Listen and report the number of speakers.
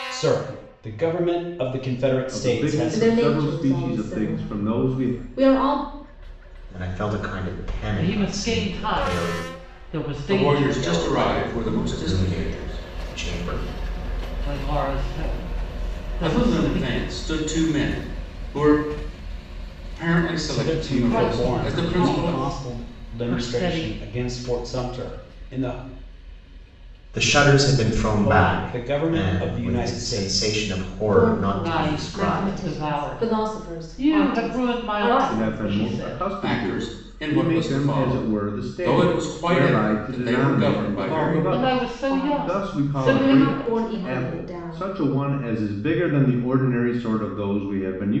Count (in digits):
6